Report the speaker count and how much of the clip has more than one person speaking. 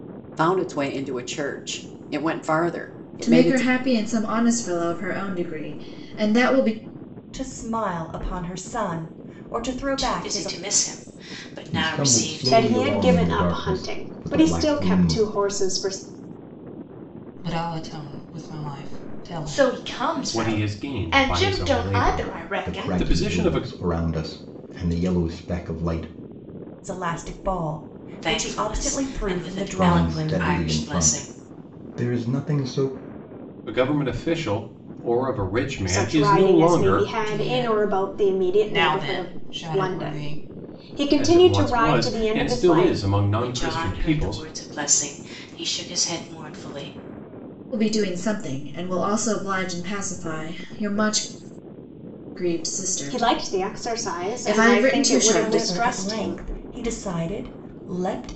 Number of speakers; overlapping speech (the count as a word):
nine, about 39%